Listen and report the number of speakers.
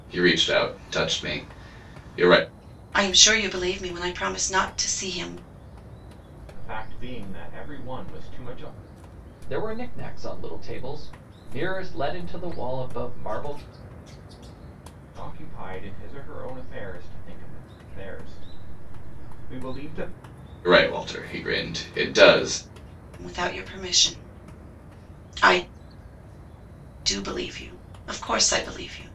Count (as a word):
four